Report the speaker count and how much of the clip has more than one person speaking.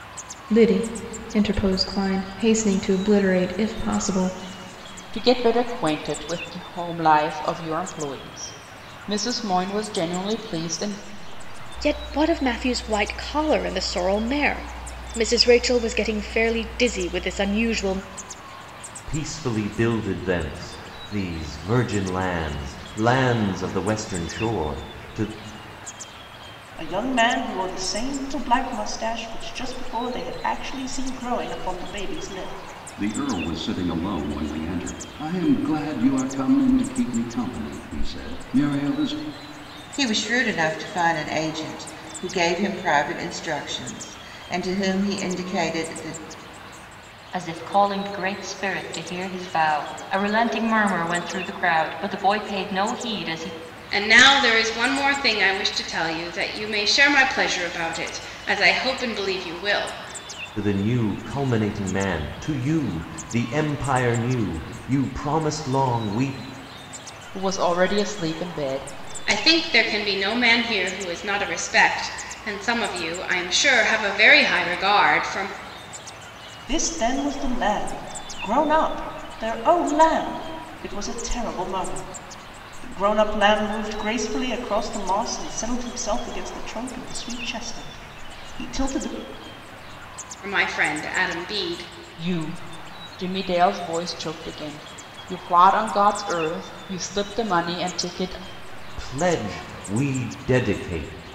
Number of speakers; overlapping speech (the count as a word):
nine, no overlap